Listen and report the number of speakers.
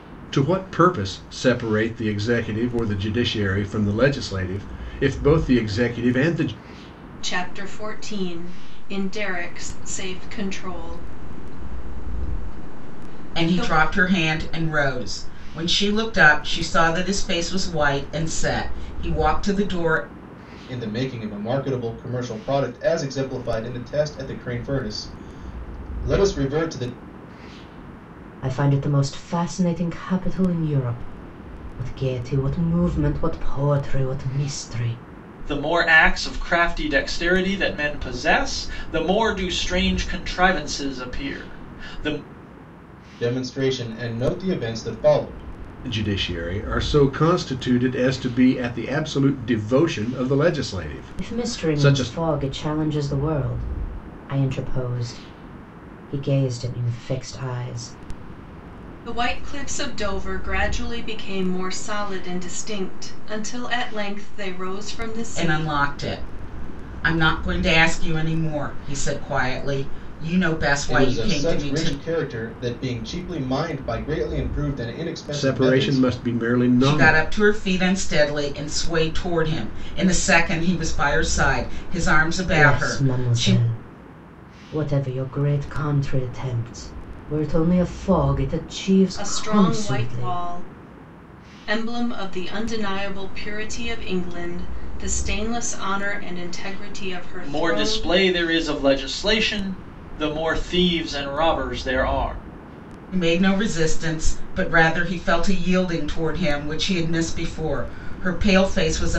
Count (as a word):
six